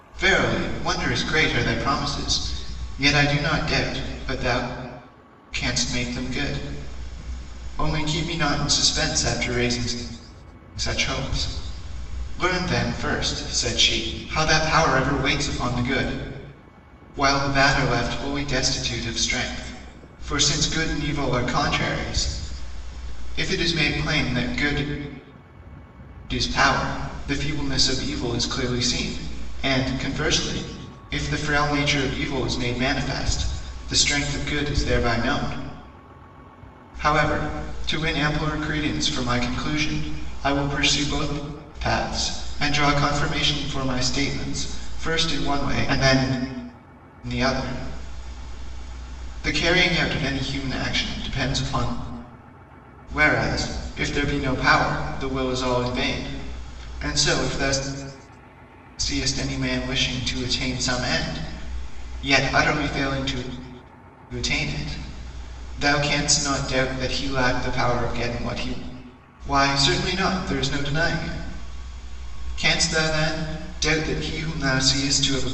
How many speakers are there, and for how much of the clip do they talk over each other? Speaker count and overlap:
1, no overlap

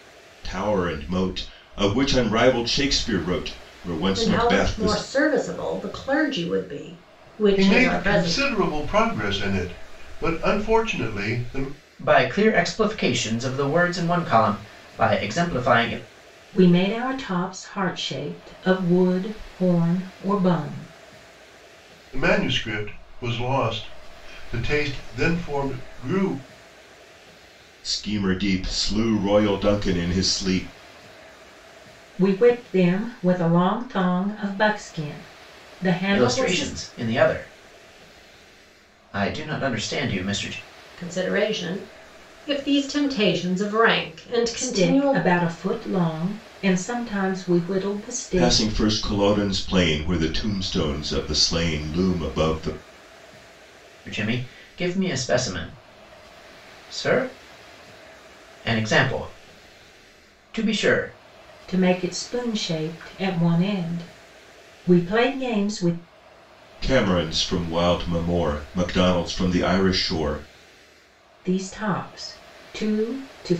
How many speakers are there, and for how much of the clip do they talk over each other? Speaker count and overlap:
5, about 5%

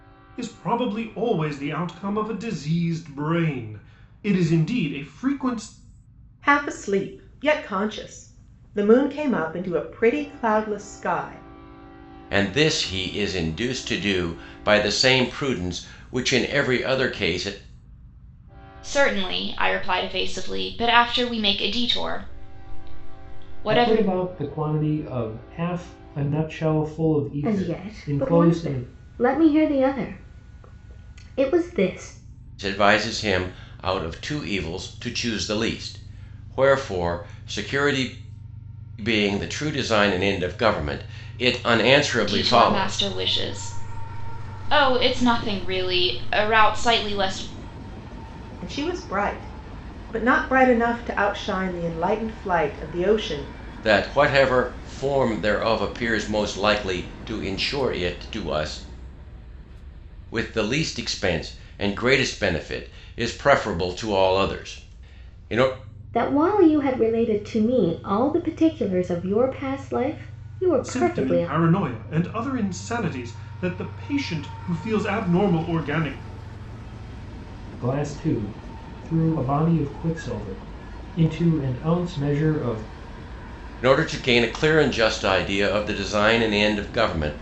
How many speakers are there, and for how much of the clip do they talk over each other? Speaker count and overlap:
6, about 4%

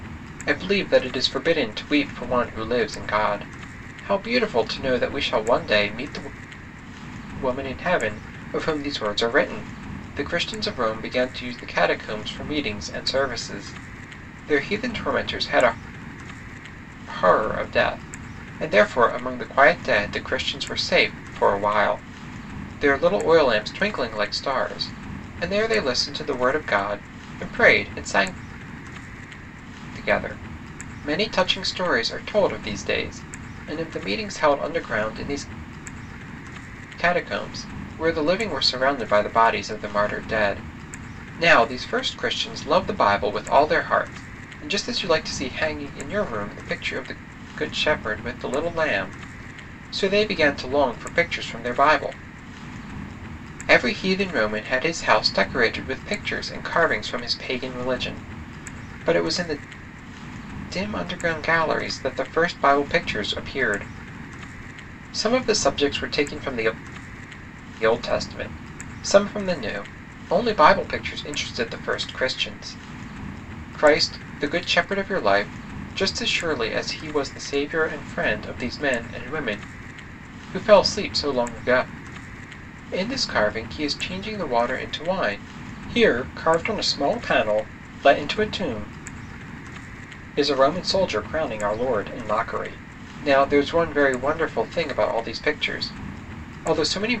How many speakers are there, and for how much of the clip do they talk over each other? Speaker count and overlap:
1, no overlap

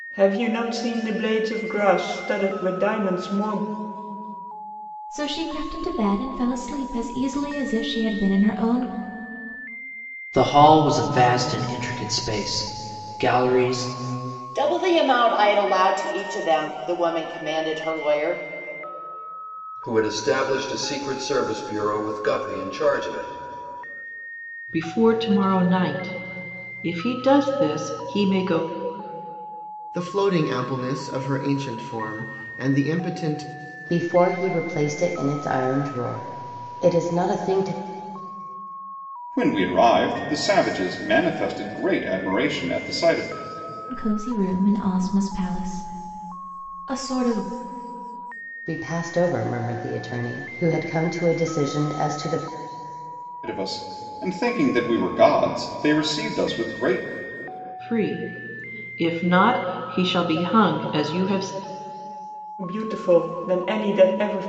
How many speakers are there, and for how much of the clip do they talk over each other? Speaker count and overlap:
9, no overlap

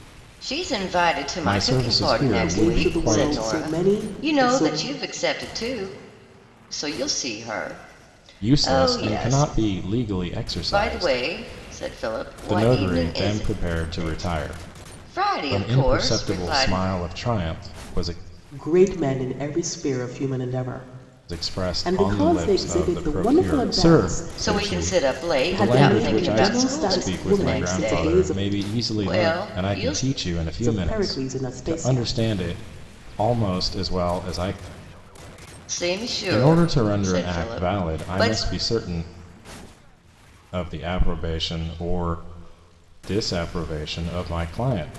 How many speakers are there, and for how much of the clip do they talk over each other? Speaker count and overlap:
3, about 44%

